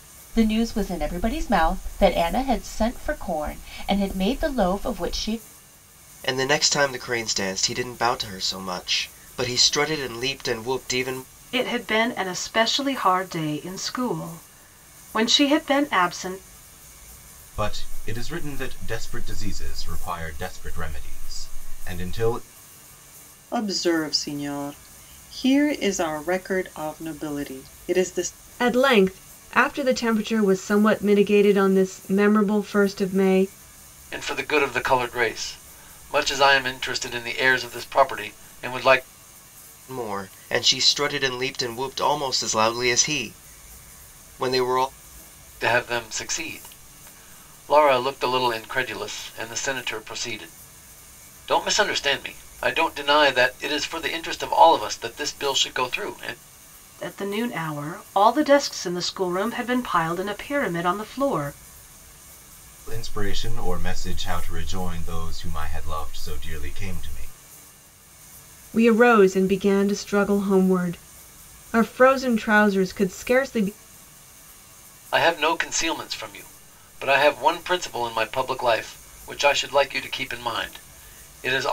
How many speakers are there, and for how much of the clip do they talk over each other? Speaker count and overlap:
seven, no overlap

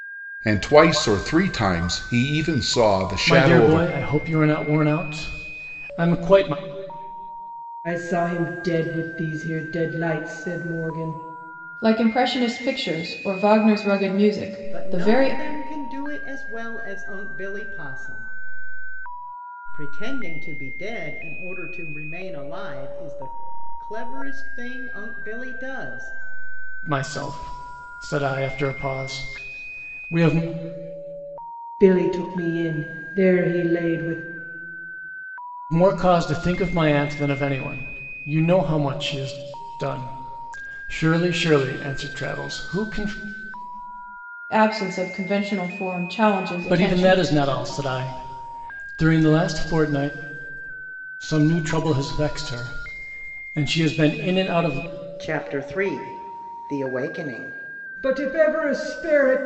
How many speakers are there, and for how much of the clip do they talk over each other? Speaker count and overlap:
five, about 3%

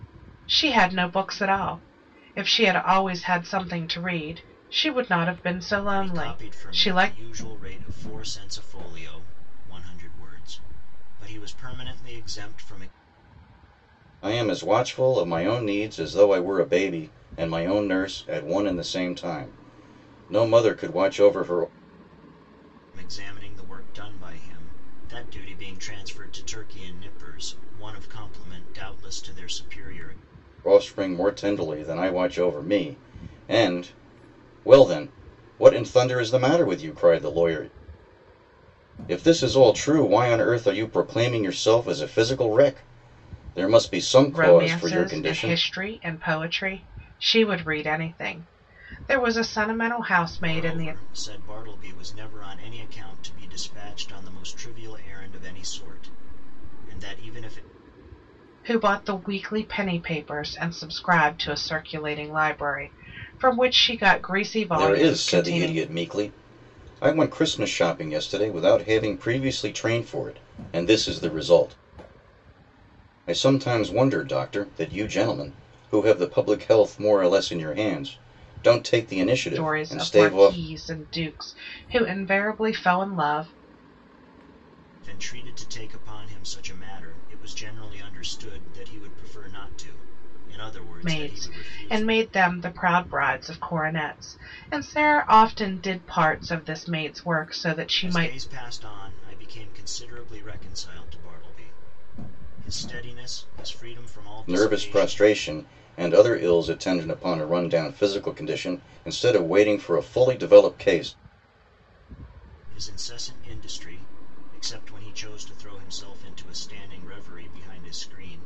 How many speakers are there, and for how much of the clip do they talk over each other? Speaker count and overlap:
three, about 7%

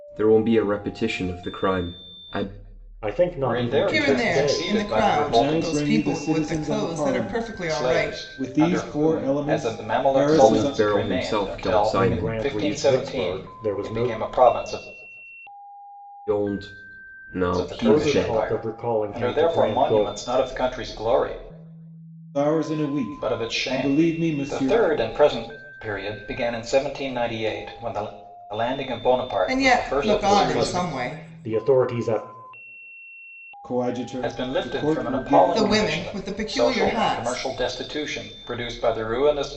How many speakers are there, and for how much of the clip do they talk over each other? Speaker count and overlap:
five, about 49%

